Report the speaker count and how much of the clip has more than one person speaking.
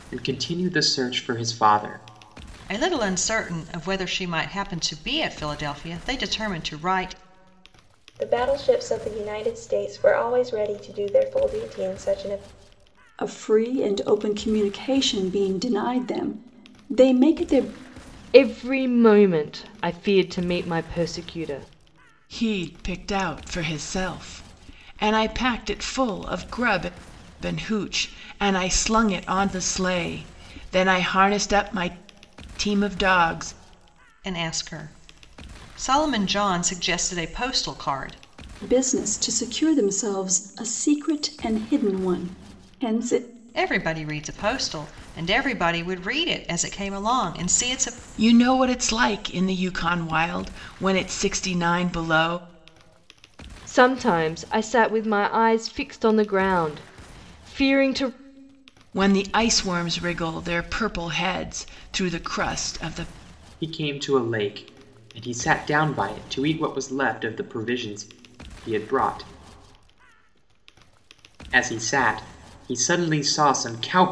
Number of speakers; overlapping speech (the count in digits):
6, no overlap